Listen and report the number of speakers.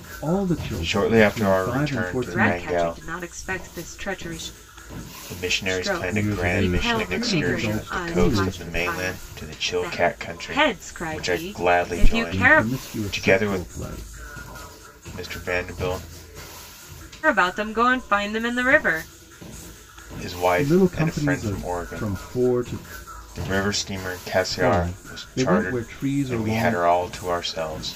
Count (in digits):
3